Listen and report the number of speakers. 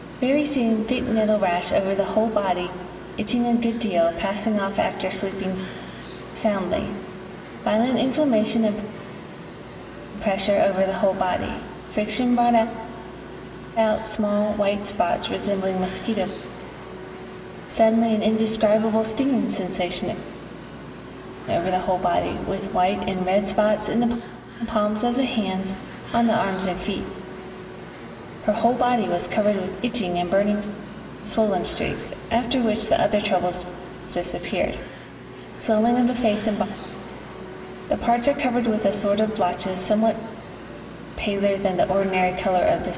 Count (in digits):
1